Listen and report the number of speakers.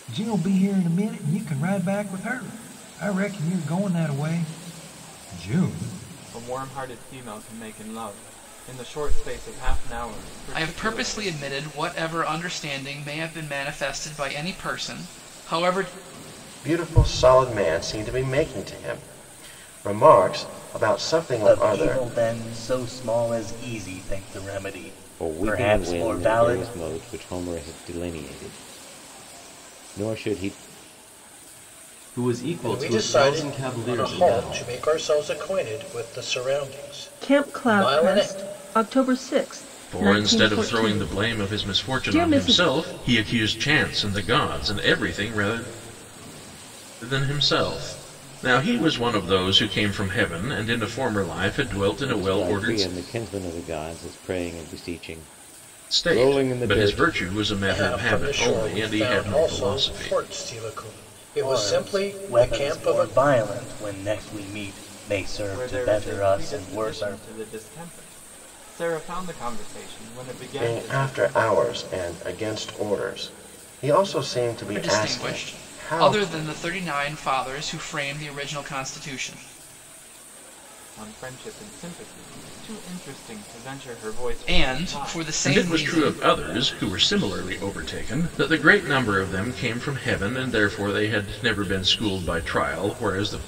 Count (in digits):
10